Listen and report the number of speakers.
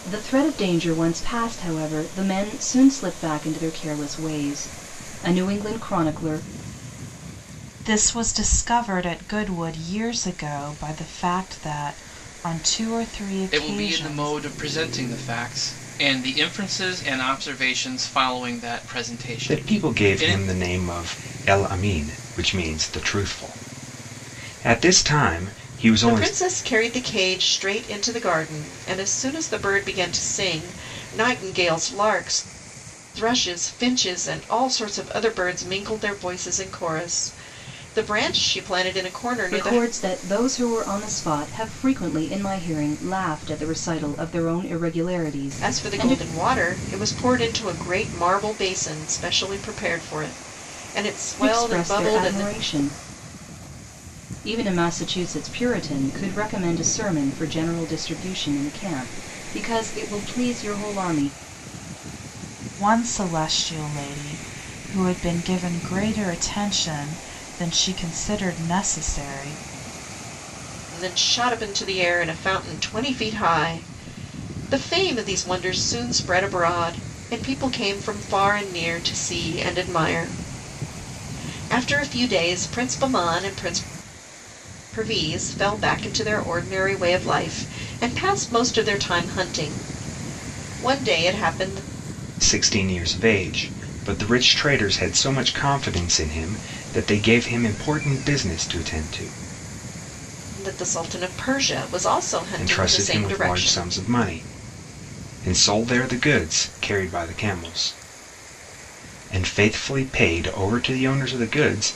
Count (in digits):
5